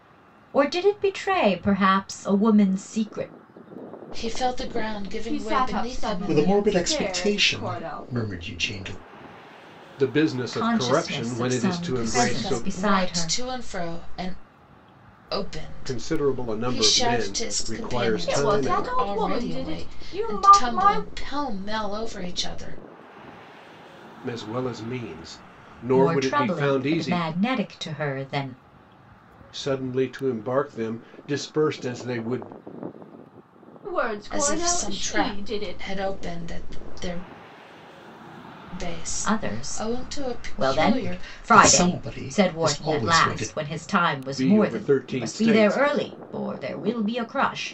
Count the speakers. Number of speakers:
five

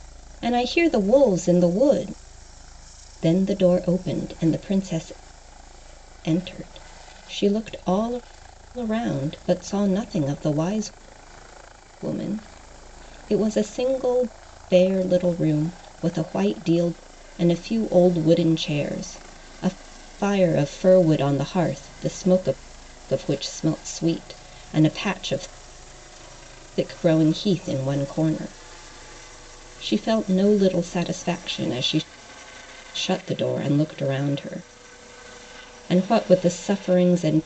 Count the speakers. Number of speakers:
one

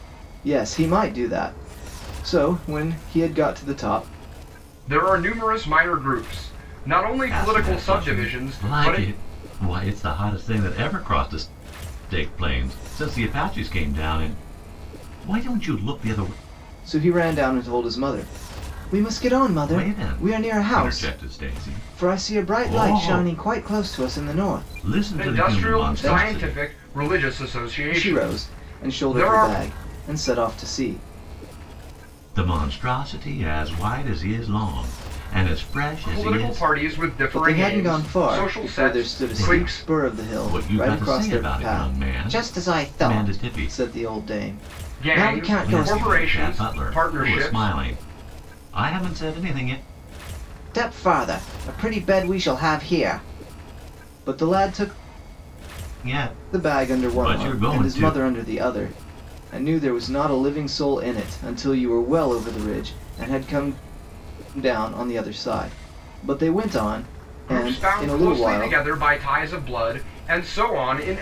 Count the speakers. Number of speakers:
three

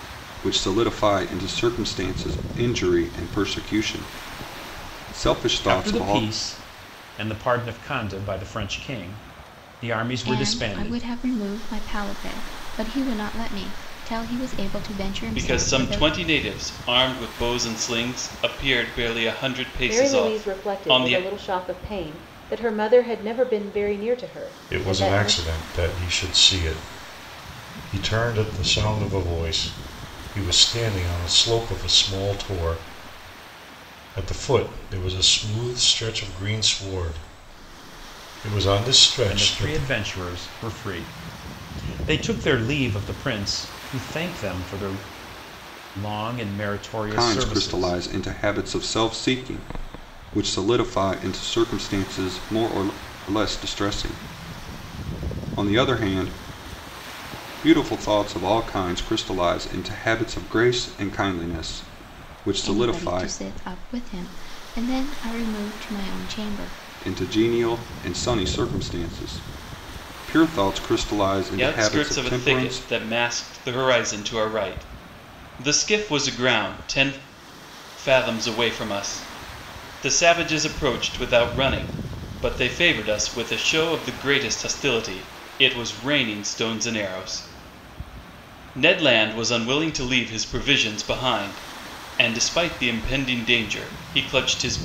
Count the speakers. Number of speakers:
six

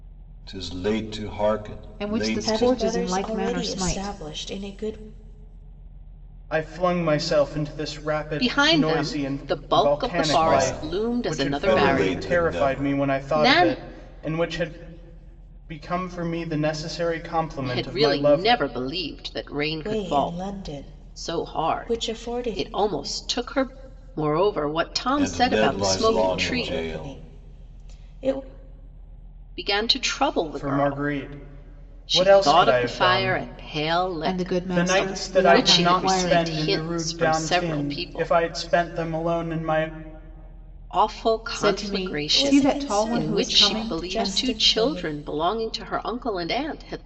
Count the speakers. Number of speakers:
five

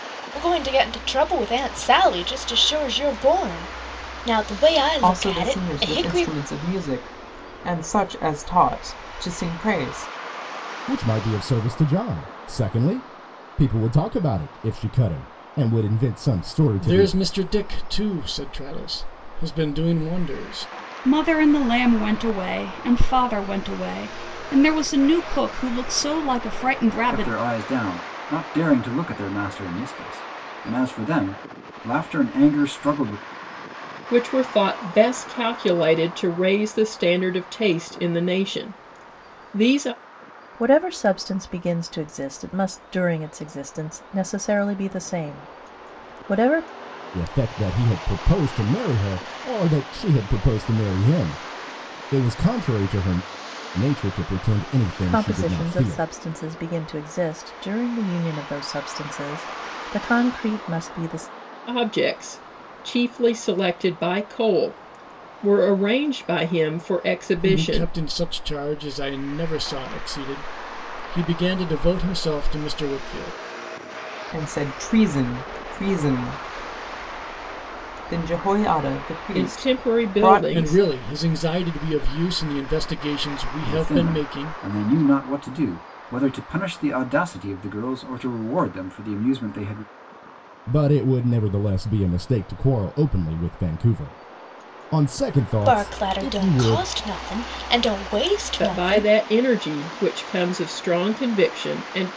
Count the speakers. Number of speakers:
eight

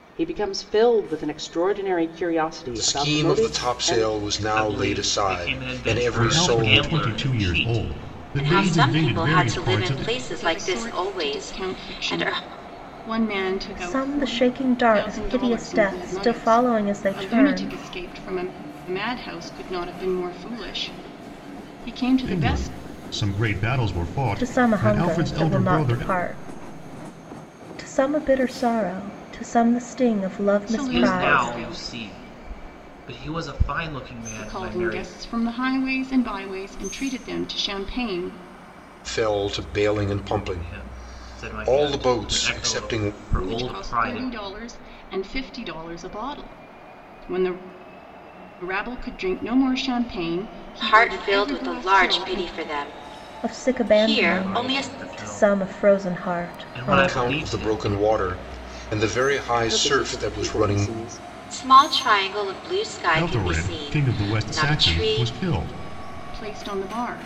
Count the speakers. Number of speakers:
seven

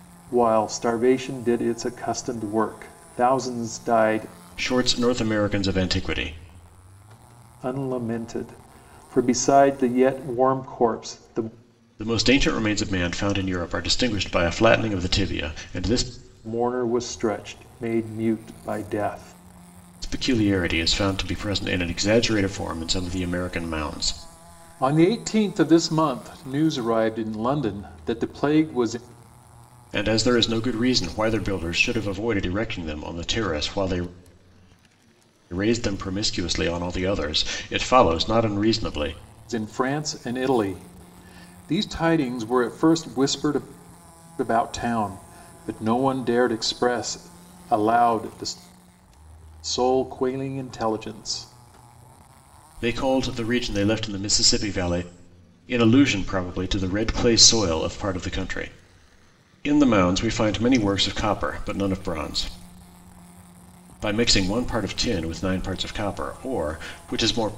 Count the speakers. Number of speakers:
two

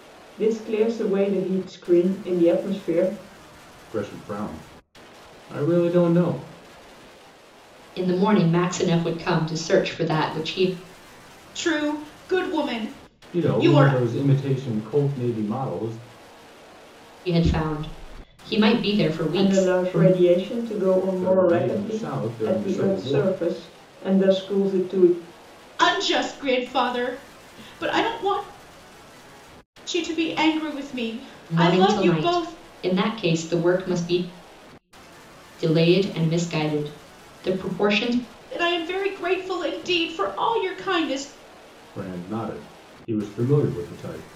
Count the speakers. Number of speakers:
four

